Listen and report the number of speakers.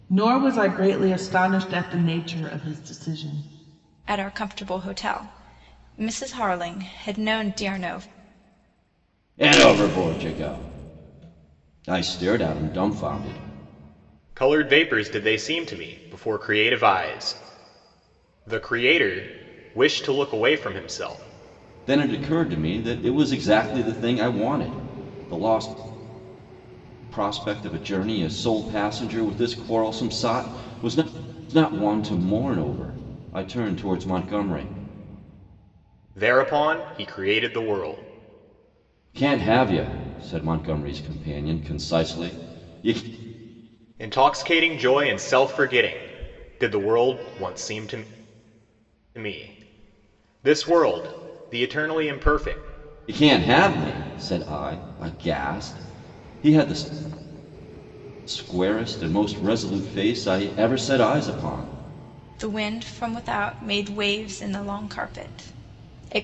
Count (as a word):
four